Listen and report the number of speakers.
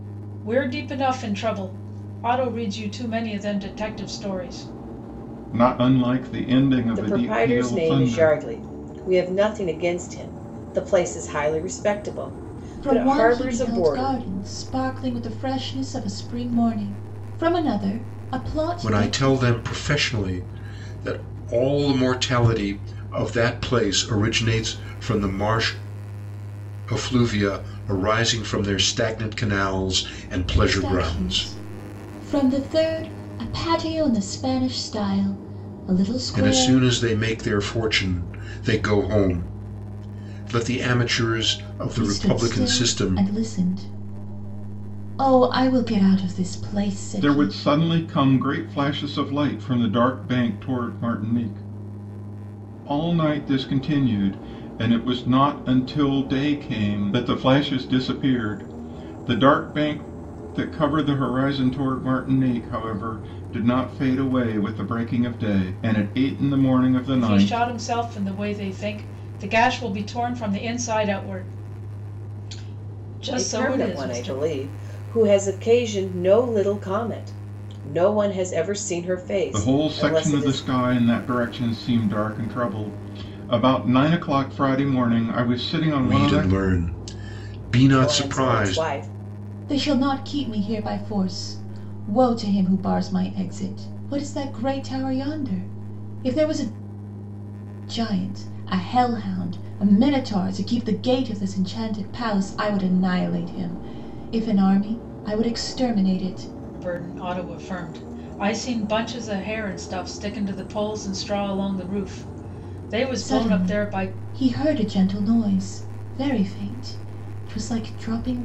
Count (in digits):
5